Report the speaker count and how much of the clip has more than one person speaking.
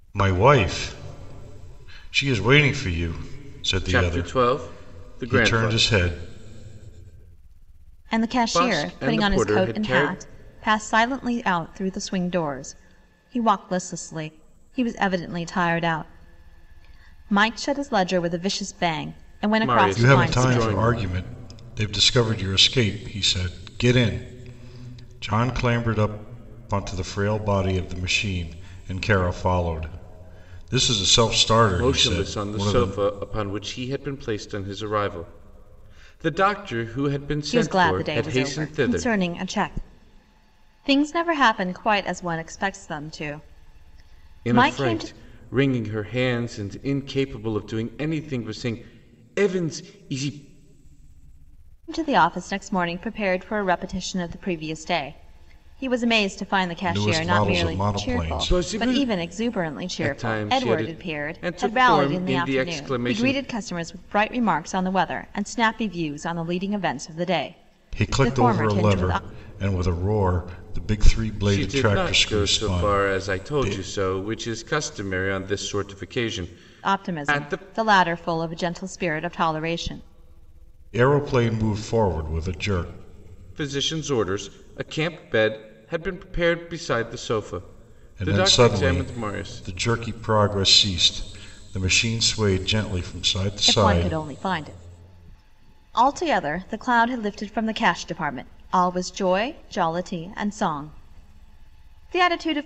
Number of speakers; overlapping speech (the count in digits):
3, about 22%